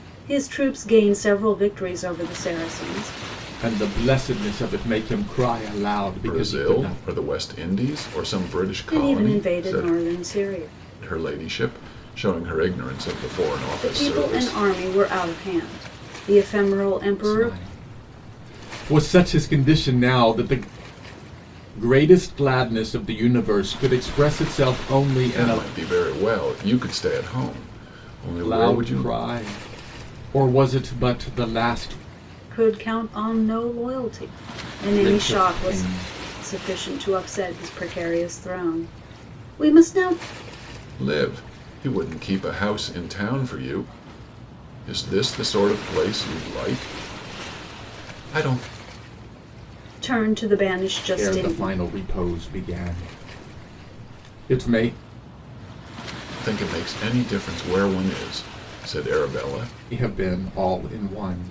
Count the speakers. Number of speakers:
three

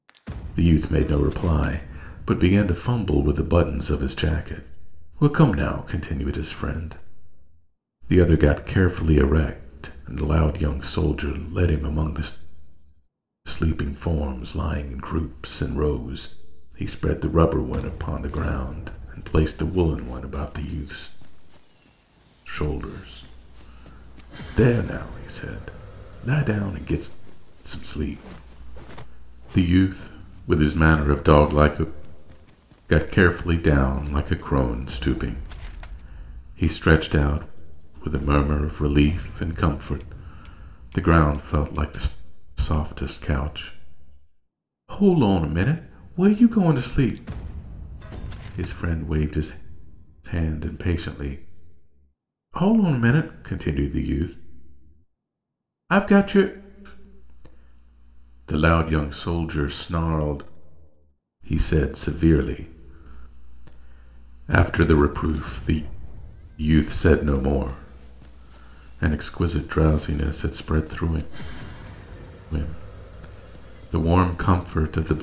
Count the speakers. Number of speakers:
one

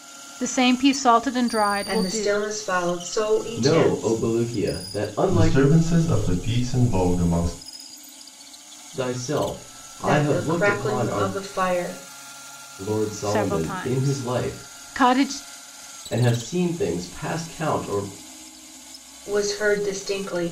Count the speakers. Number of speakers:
four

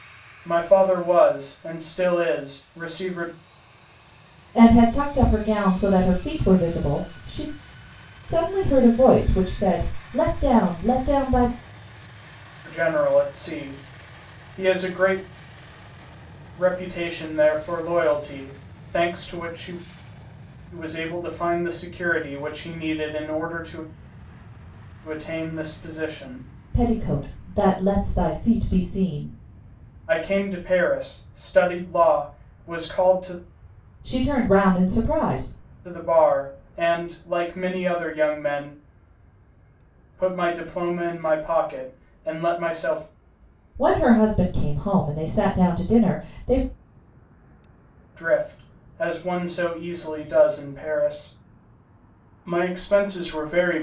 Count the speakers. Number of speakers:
two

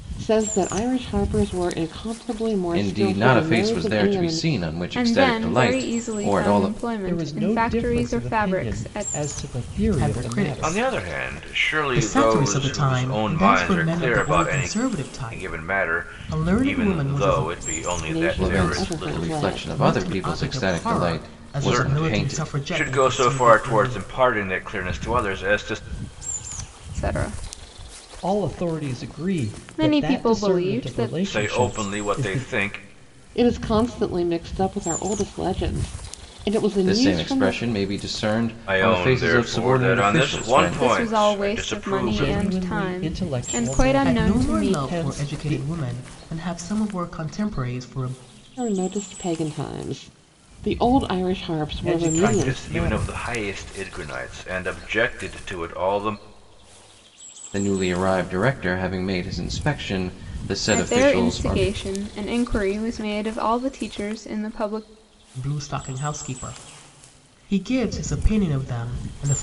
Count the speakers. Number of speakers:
six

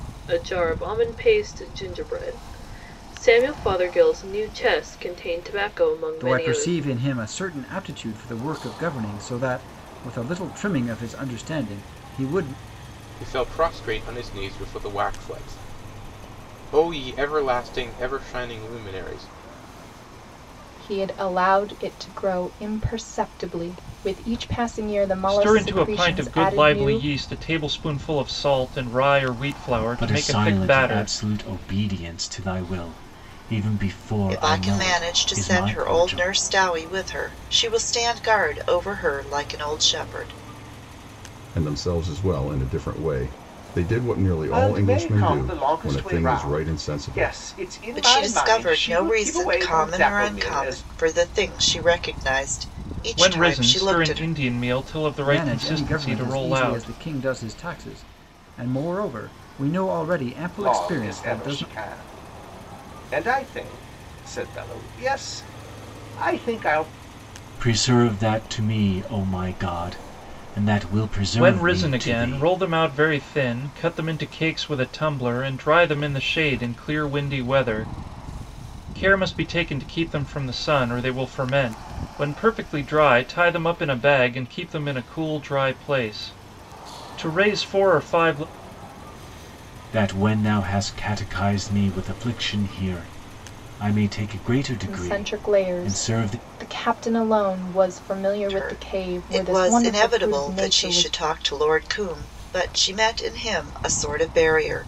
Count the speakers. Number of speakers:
nine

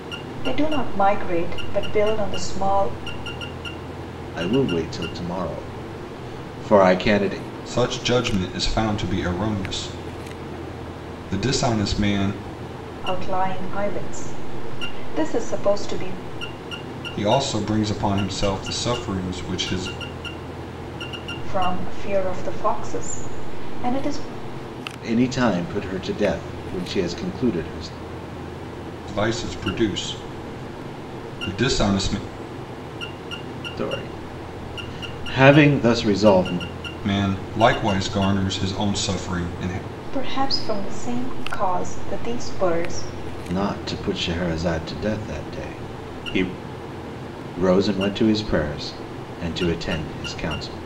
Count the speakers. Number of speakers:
three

